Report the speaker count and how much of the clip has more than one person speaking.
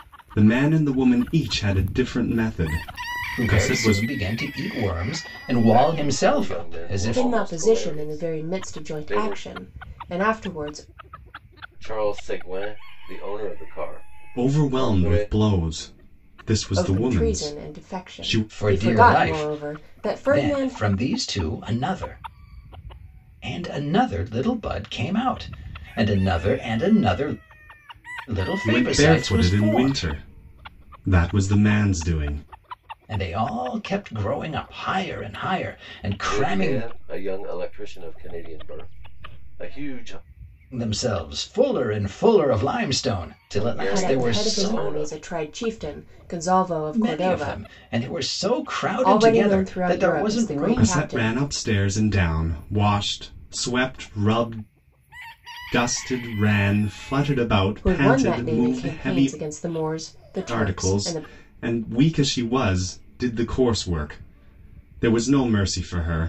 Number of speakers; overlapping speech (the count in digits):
4, about 28%